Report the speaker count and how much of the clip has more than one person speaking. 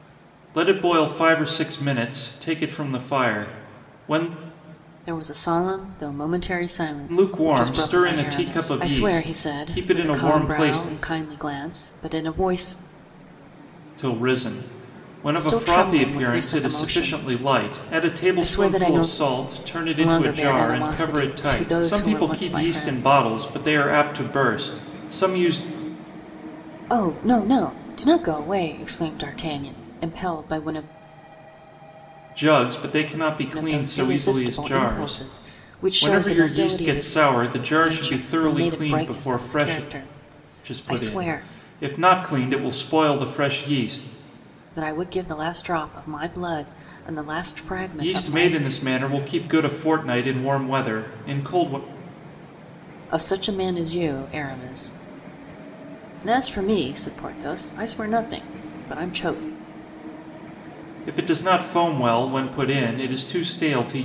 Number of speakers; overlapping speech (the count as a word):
two, about 27%